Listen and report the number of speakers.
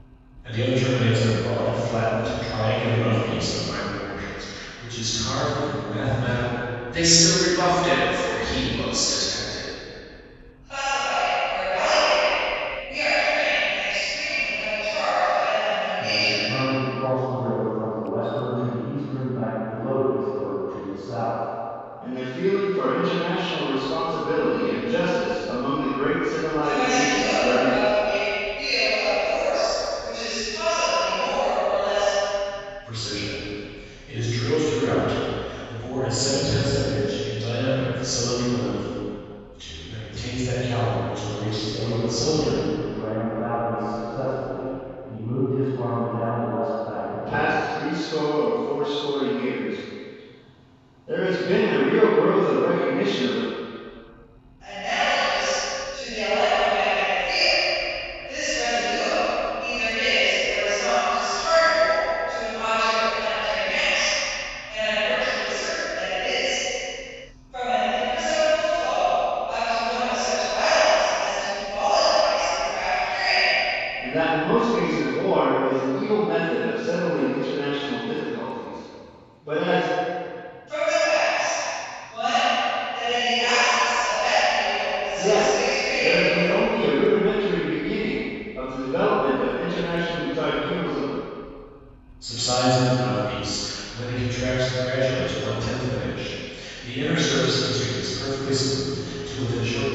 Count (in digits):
5